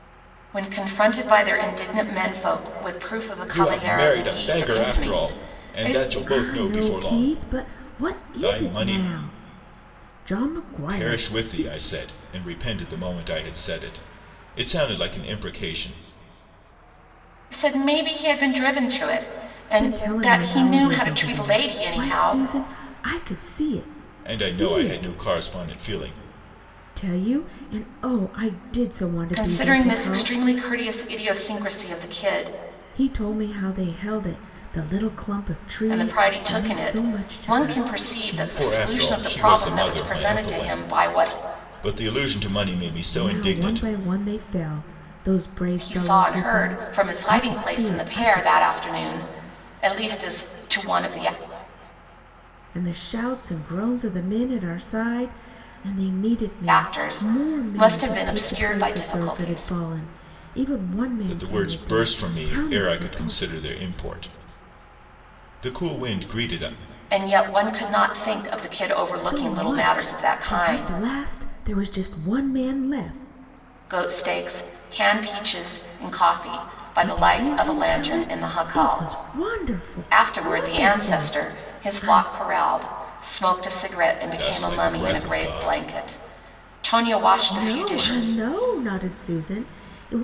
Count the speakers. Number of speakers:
3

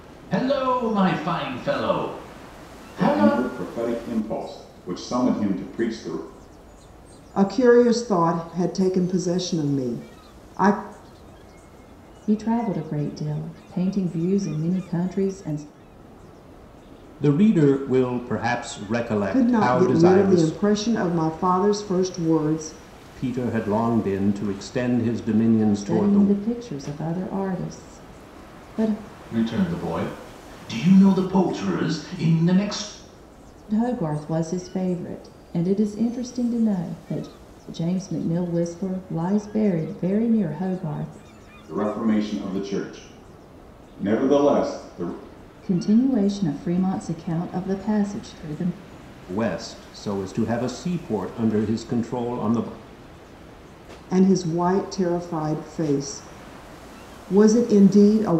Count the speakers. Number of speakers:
5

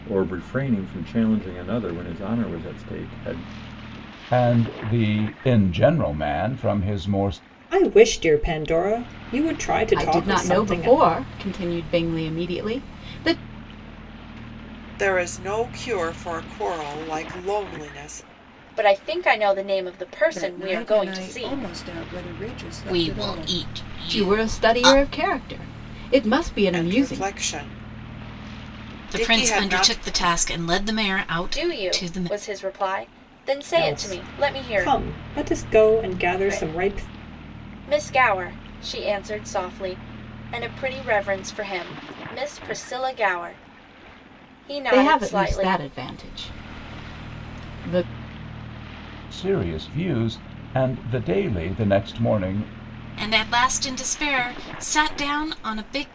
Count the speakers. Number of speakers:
8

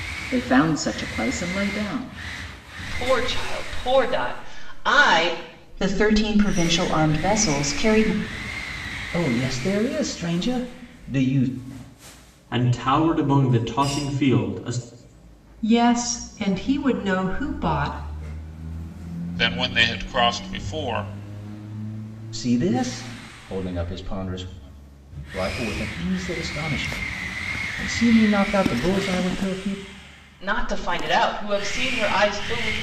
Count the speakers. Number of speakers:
7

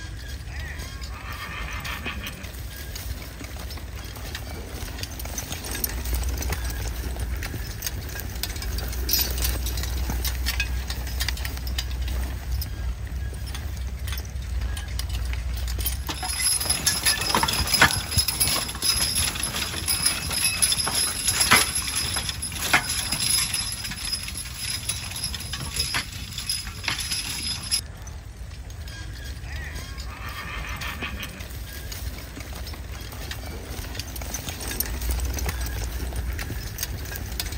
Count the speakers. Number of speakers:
0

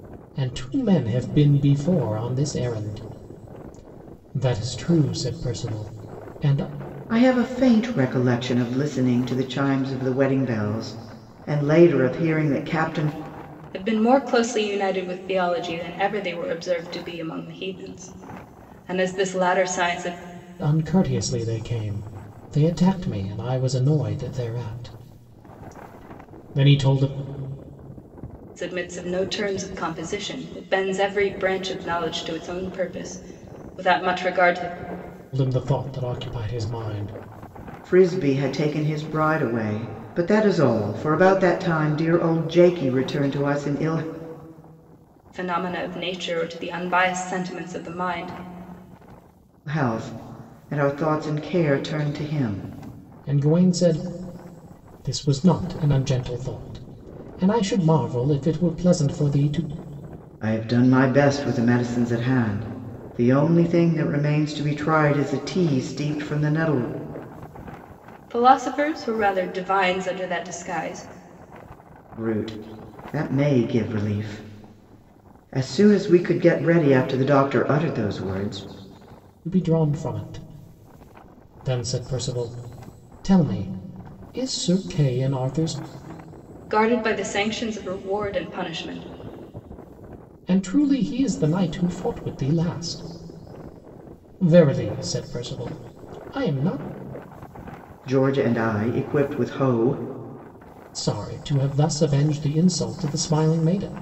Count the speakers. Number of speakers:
3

